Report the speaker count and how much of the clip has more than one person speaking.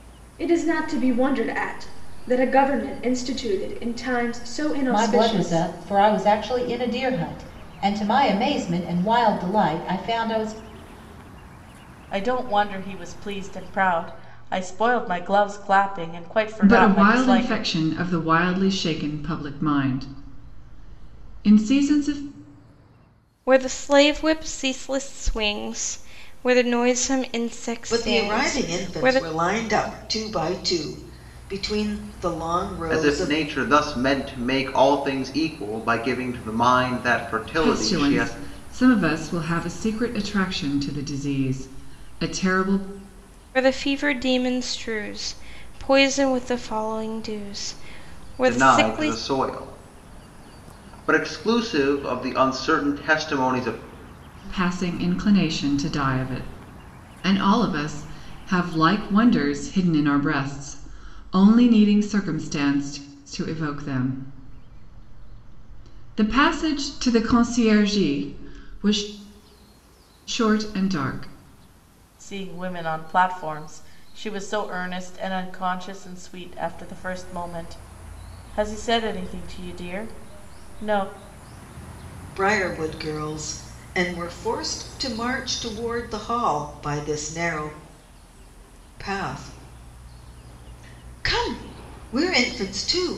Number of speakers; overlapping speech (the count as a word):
seven, about 6%